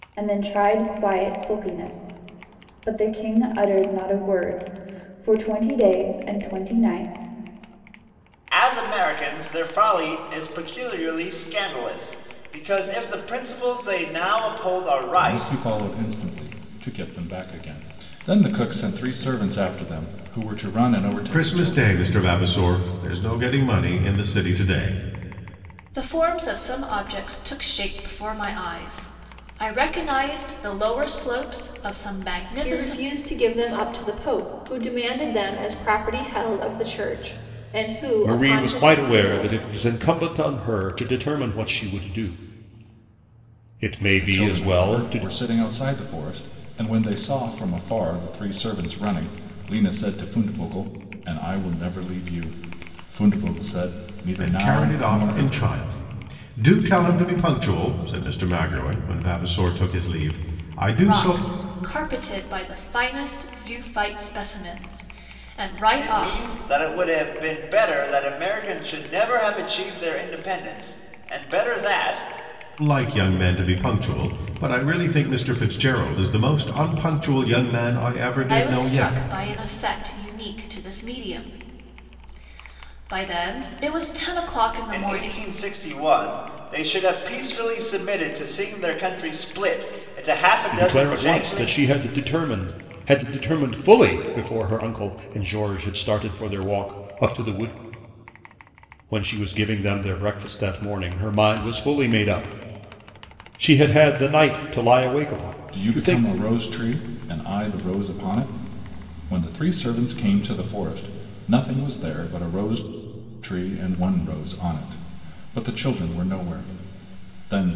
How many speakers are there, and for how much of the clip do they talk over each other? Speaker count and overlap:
7, about 8%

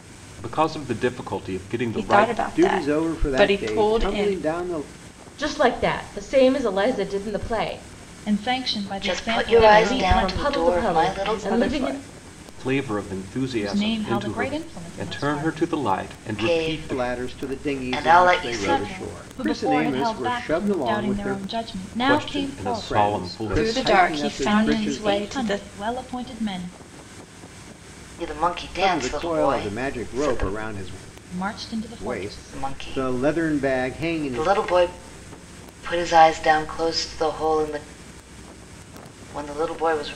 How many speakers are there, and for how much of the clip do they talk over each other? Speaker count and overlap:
6, about 51%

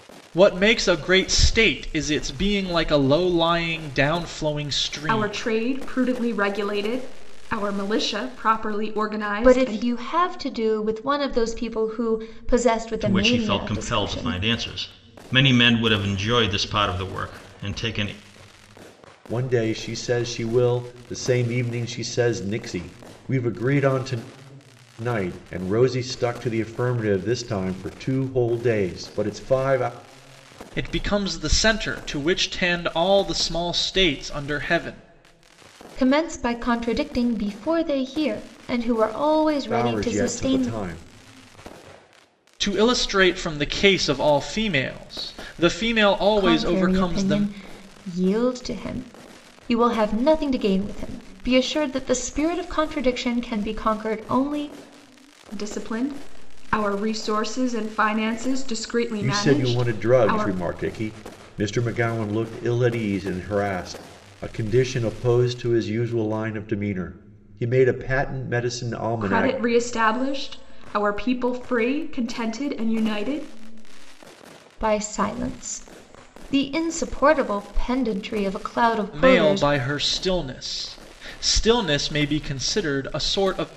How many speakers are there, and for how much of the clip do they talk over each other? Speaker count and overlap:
5, about 8%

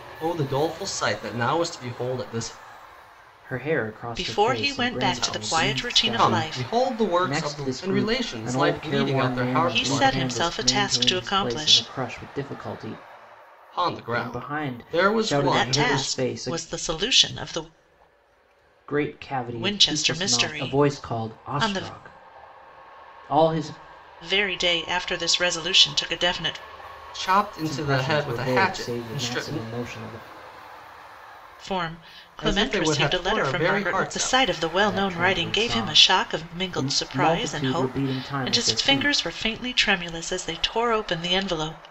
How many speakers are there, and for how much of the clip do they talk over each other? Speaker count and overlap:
3, about 49%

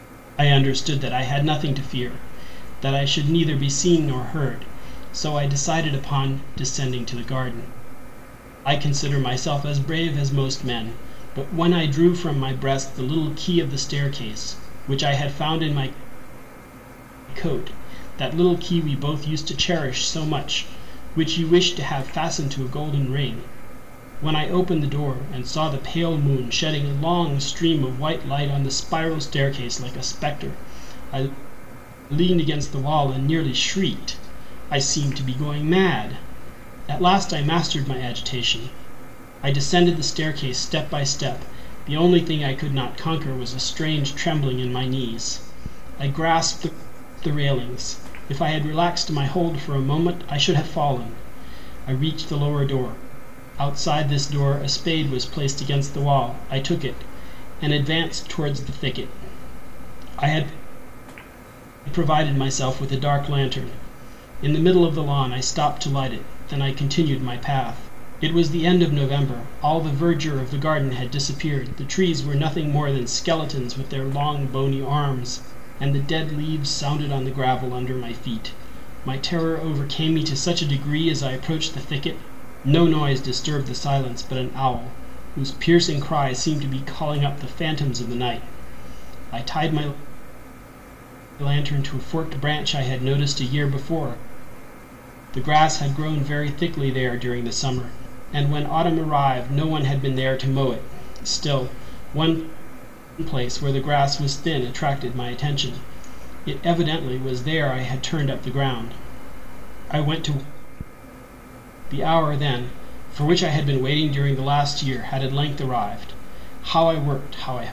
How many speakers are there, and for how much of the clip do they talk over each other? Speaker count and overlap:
1, no overlap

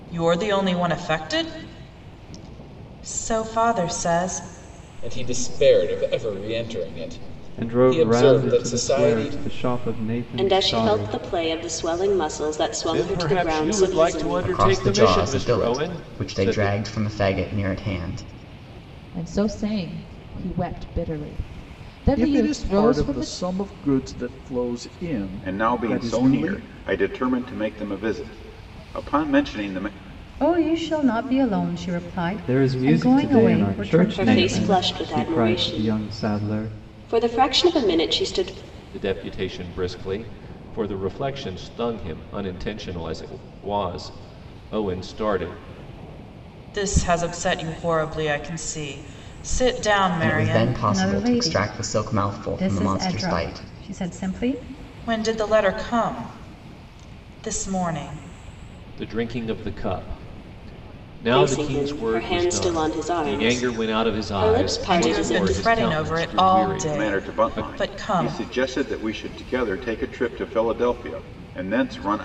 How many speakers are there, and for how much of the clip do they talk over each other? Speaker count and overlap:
10, about 33%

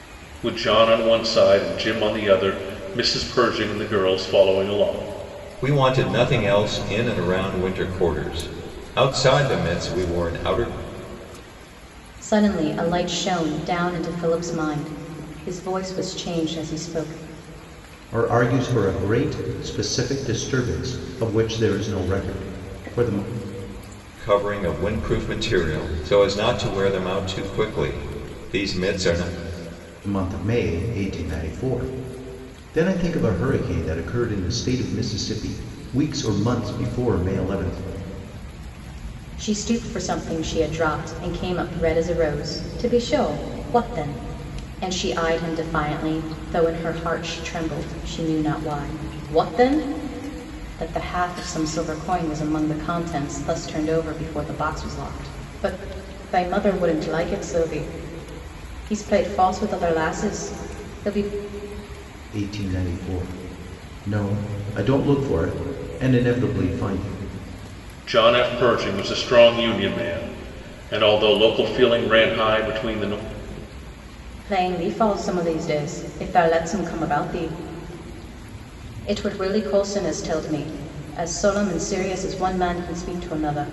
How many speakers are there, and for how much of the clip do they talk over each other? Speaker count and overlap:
4, no overlap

